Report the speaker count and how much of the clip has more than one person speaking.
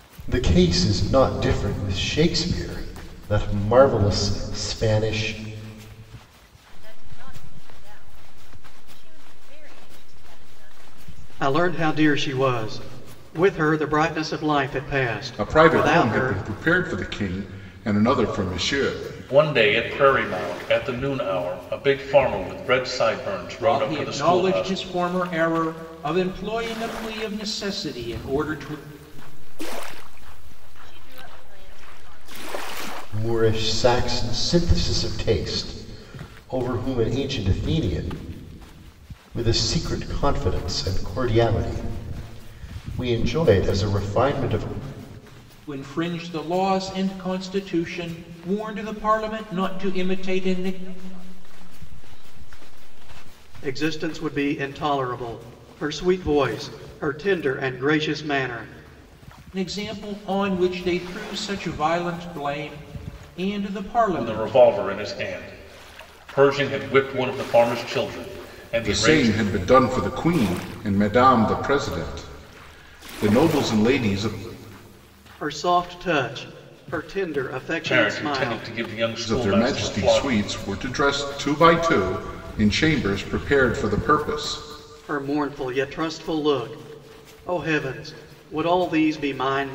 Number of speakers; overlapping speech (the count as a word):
six, about 10%